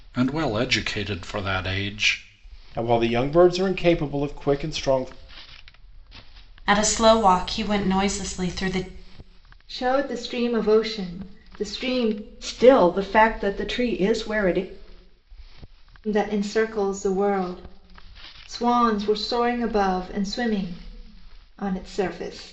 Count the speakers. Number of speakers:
5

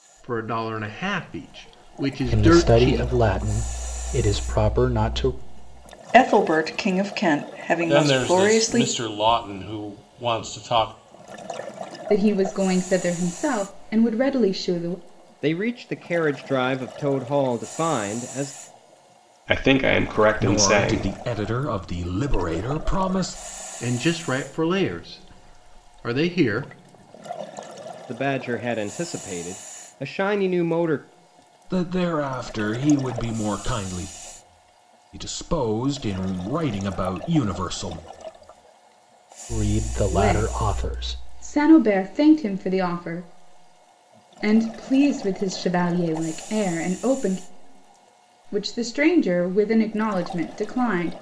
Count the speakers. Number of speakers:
8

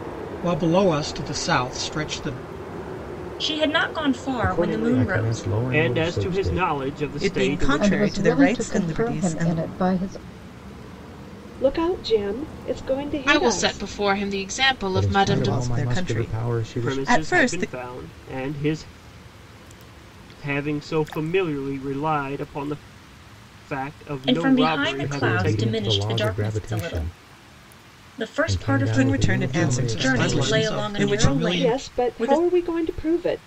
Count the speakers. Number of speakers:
8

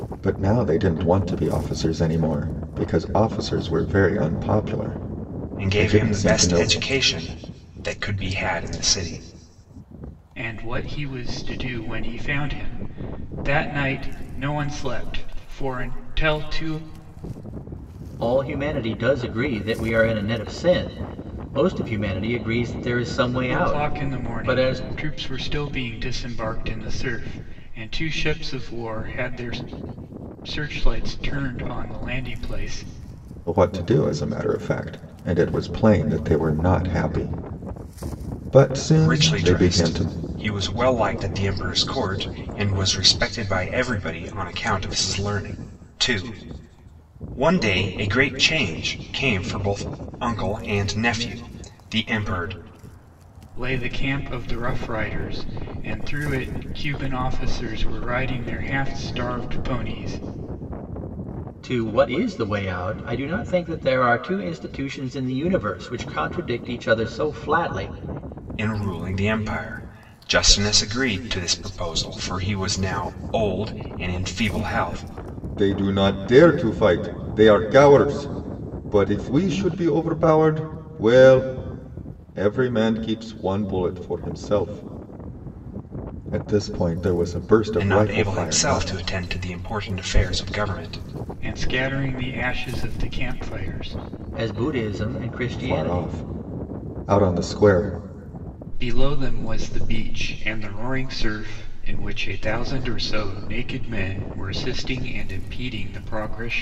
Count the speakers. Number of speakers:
4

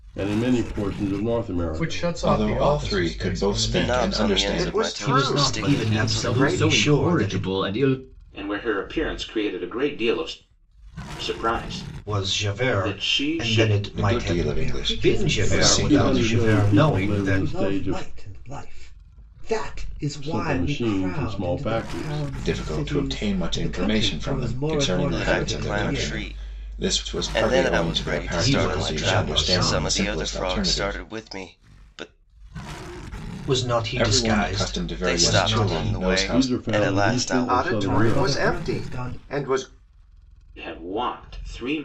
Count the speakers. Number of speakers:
9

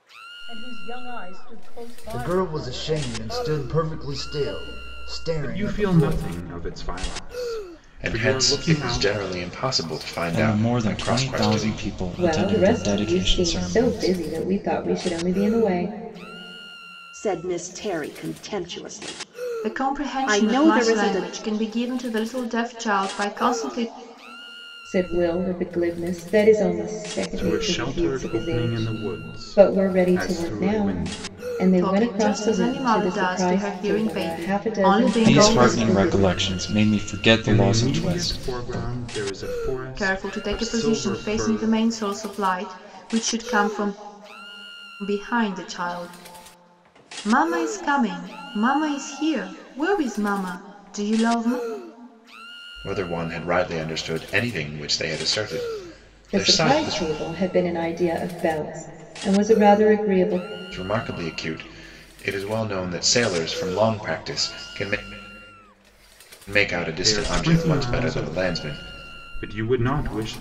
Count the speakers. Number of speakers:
8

